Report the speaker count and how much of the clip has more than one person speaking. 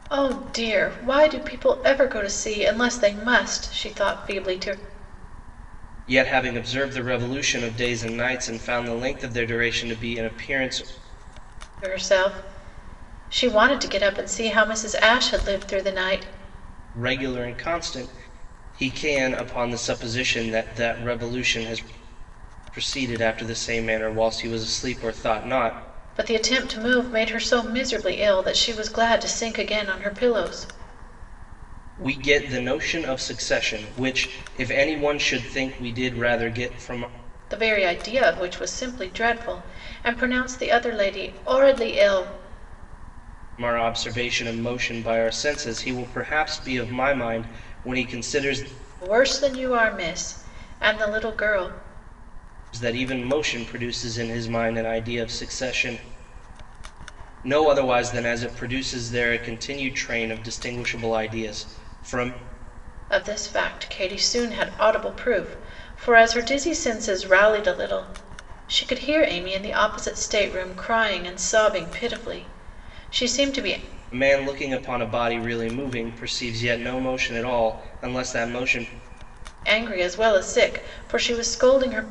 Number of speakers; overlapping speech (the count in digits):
2, no overlap